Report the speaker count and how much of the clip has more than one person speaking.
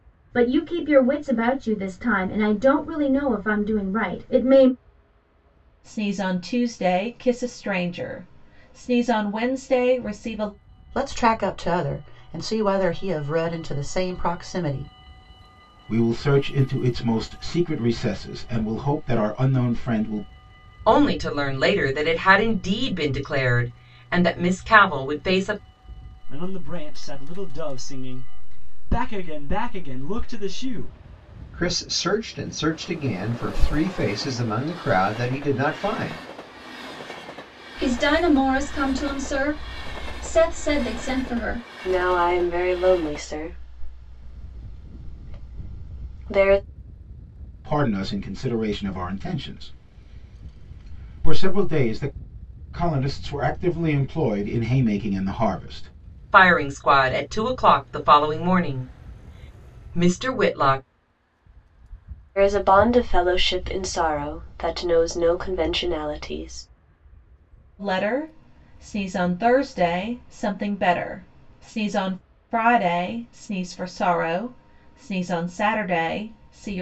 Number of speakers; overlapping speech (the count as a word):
nine, no overlap